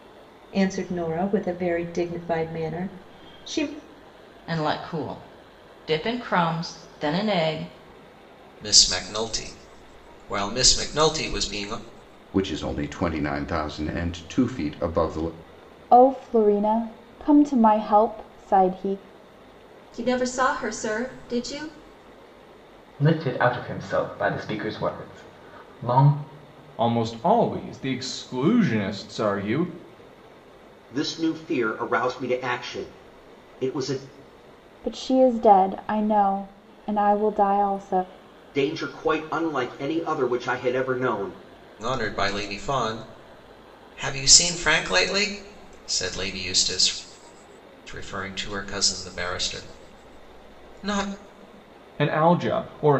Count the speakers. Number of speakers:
9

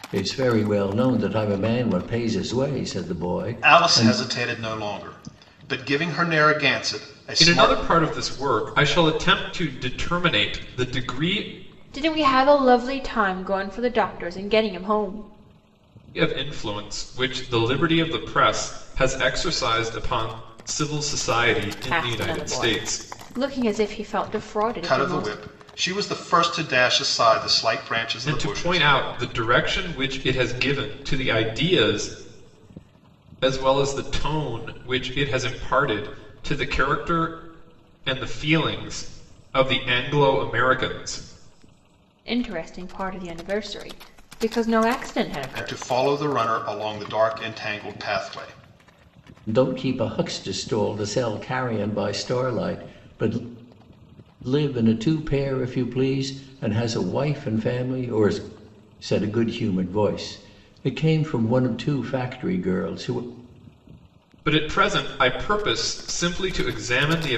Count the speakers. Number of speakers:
4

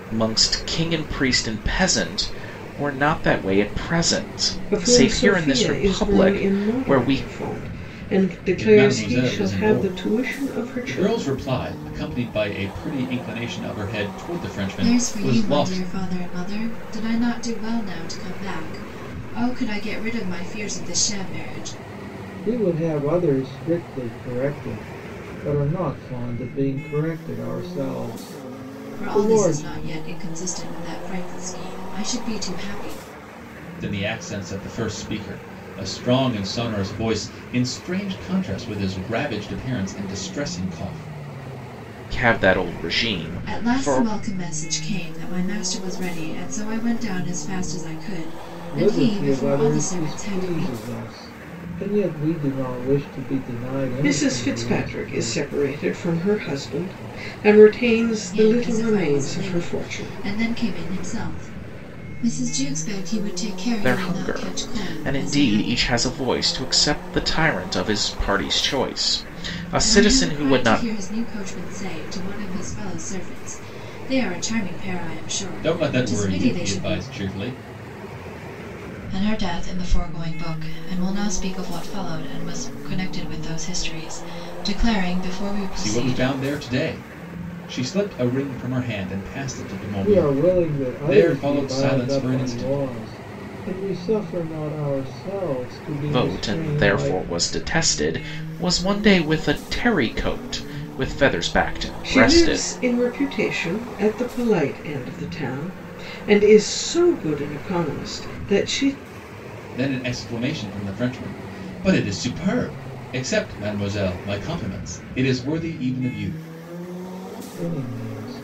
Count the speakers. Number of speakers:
5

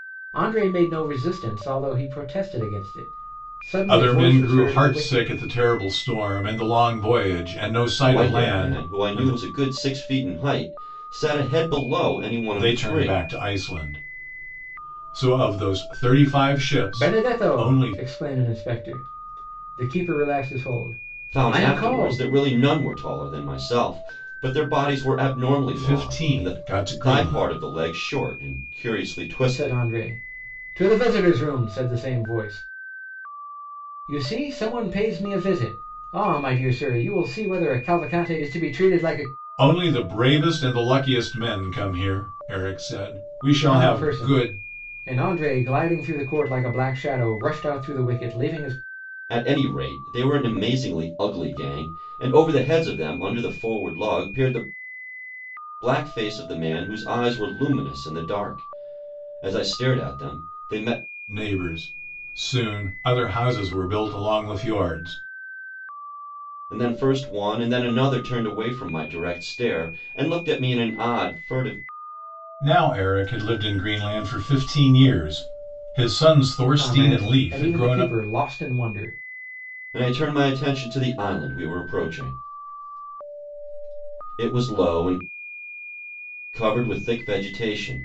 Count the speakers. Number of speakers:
3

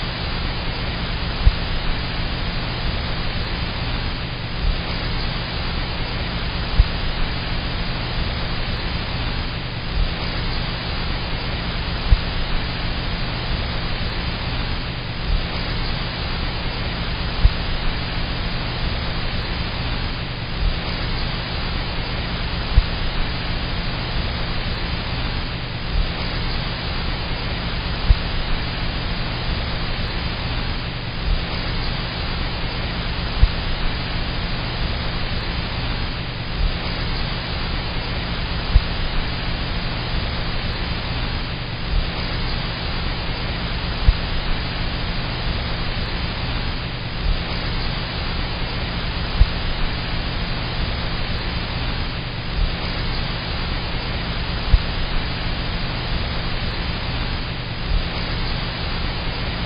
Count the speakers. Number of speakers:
0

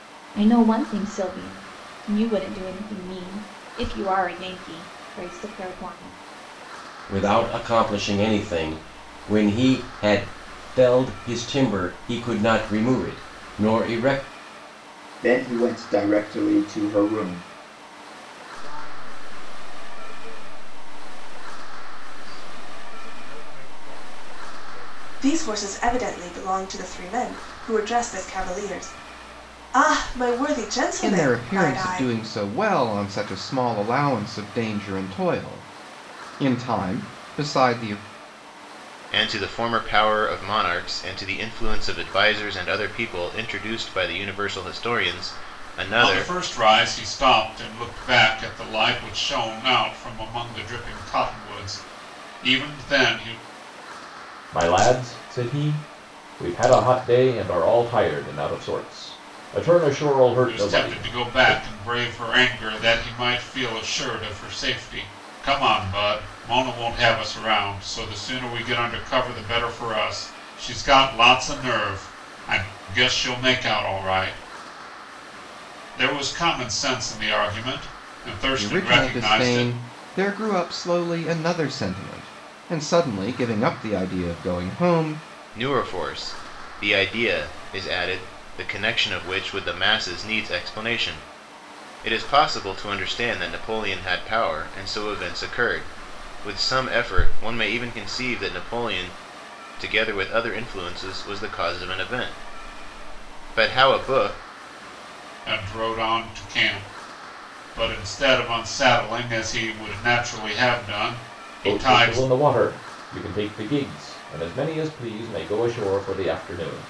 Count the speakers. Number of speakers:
9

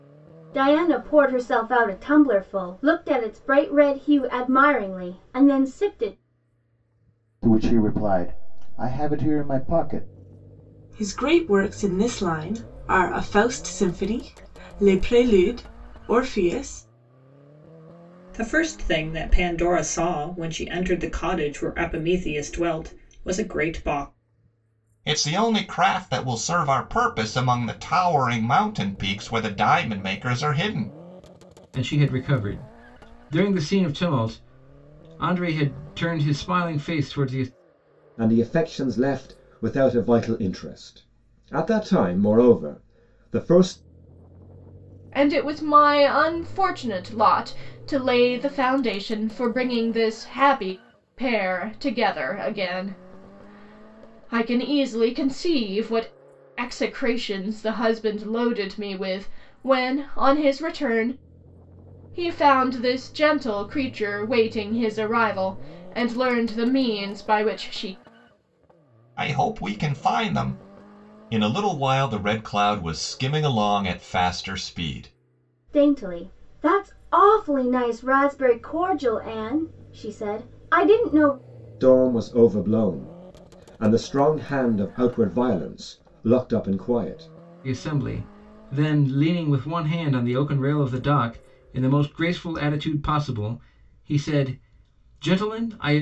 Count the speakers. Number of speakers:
8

